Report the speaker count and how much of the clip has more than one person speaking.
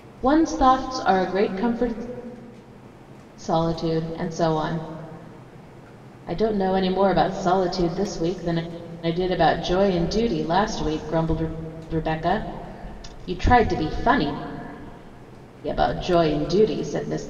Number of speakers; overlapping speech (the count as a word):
one, no overlap